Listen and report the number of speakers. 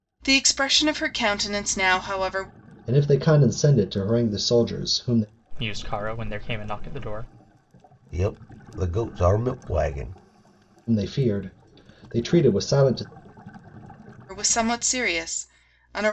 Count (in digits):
4